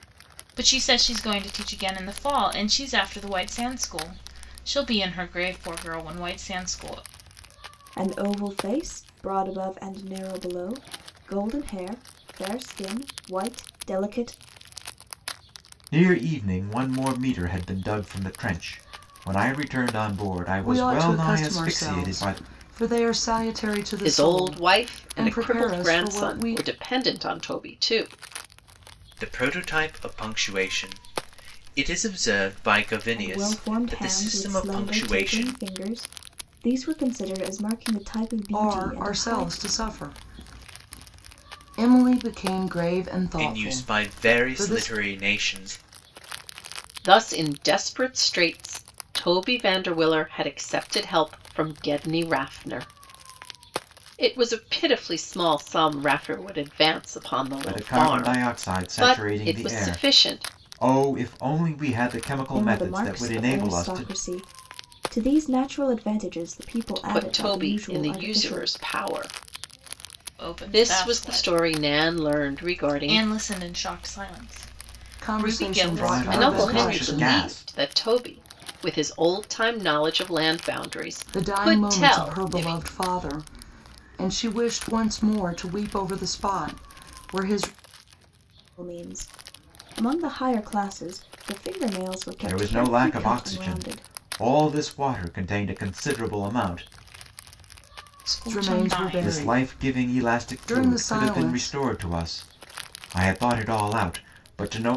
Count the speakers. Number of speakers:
six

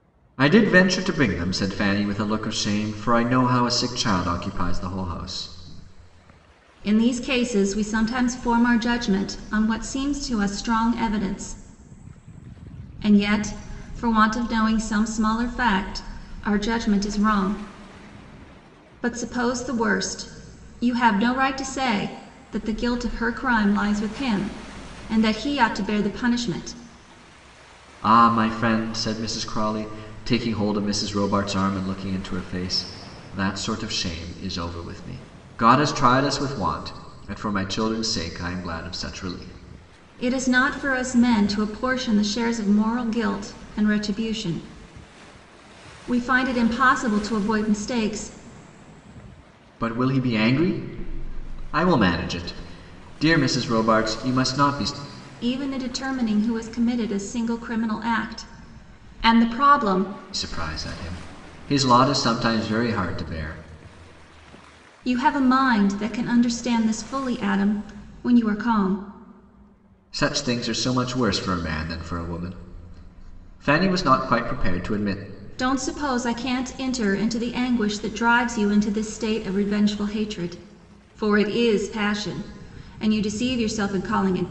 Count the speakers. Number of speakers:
two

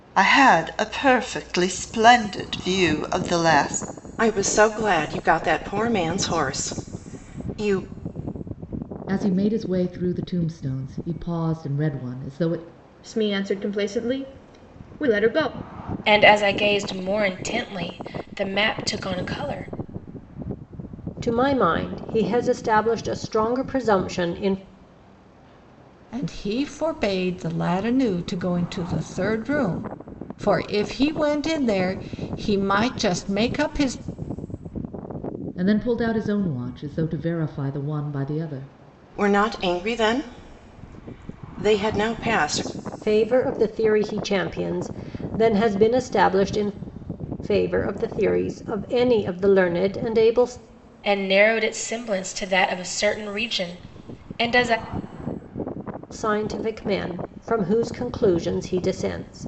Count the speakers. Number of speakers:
seven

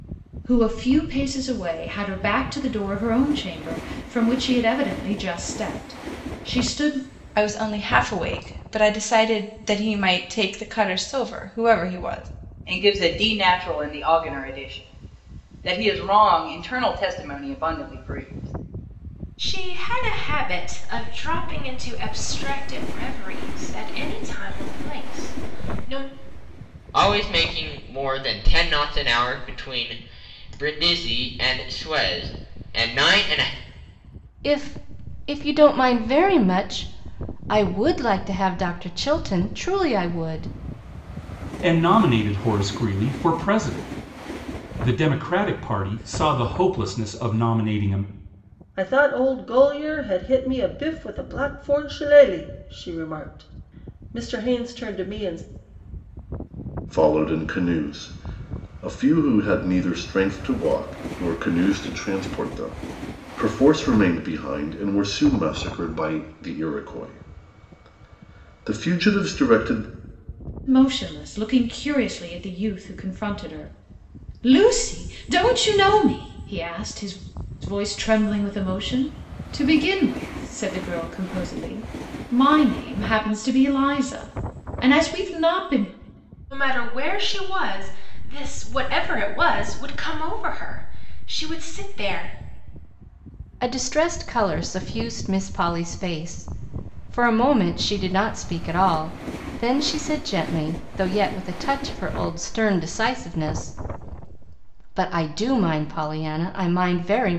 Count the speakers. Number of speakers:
nine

